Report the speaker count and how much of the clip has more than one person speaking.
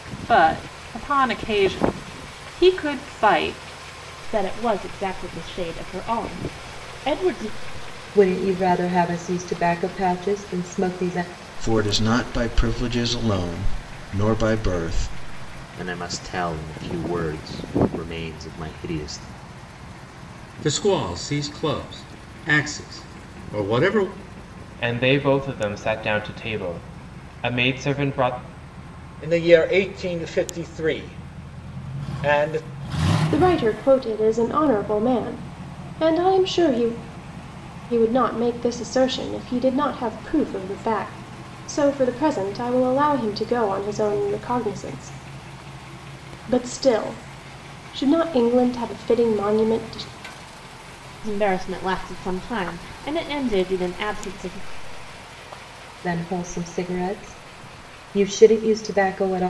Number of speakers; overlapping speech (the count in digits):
9, no overlap